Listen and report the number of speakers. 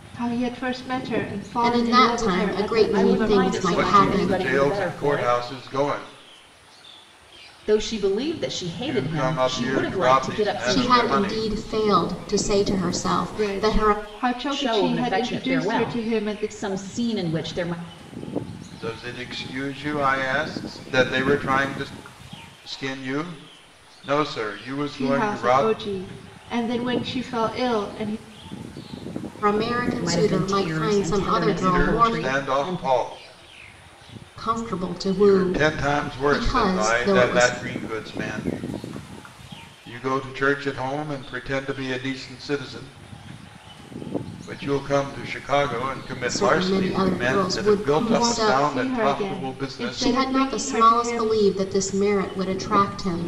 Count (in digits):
4